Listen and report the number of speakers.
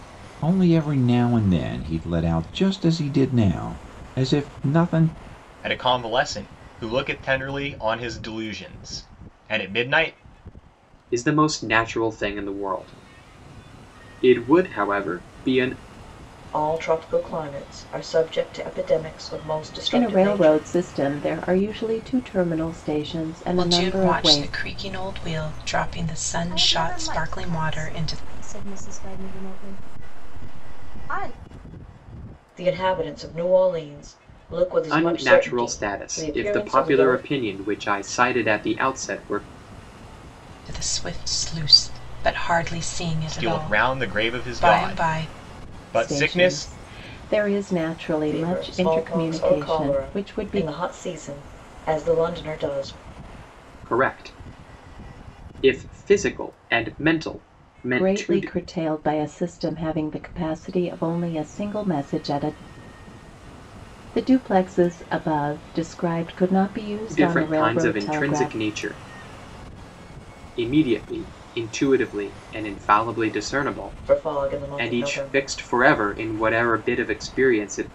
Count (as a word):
seven